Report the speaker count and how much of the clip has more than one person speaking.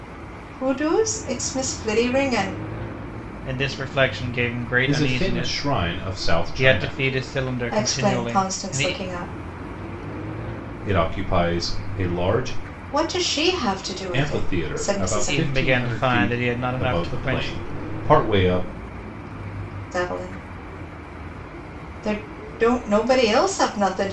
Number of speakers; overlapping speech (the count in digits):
3, about 24%